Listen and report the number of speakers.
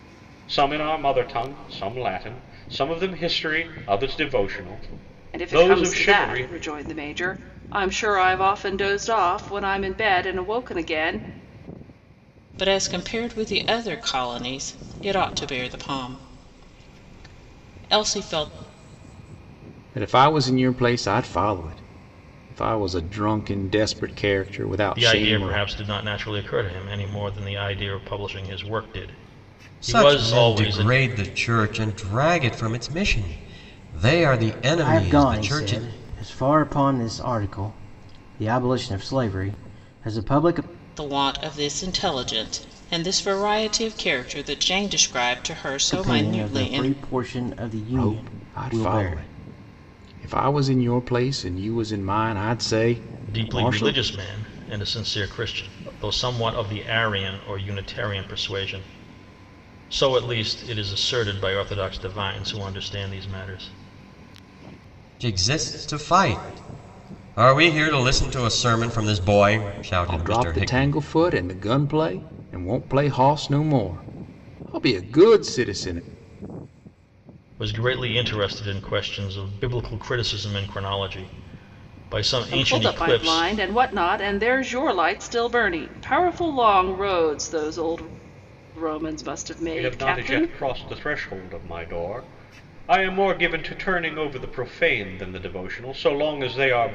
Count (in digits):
7